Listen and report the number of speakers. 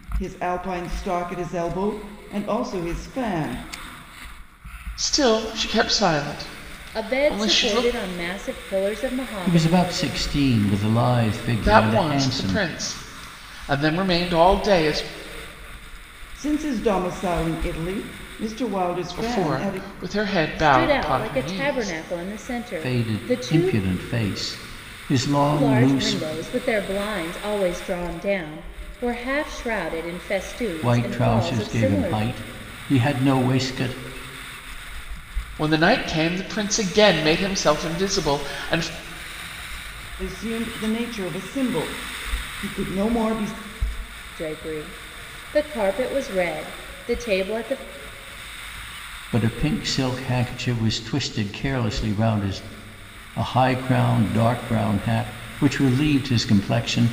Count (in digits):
4